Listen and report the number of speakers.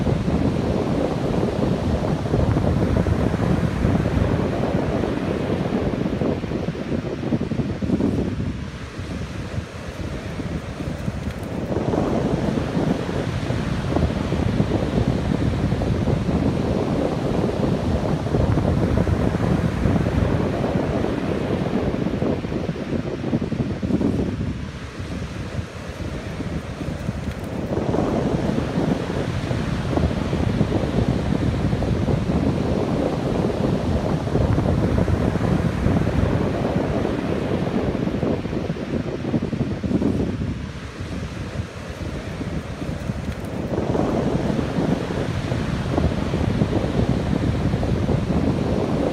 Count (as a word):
zero